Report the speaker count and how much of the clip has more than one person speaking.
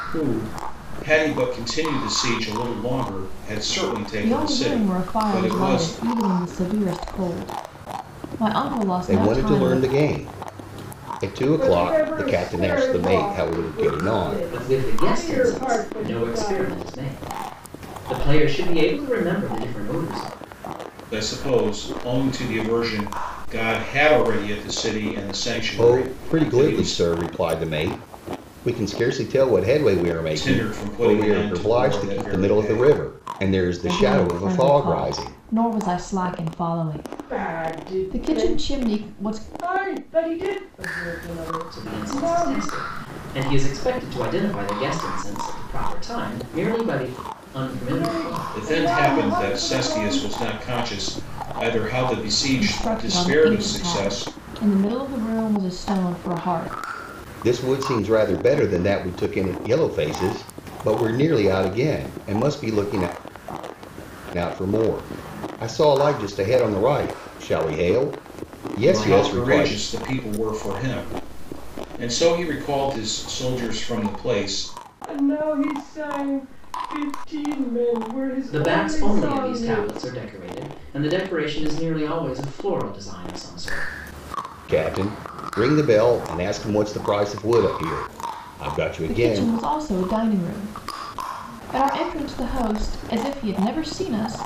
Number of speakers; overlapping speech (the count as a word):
five, about 25%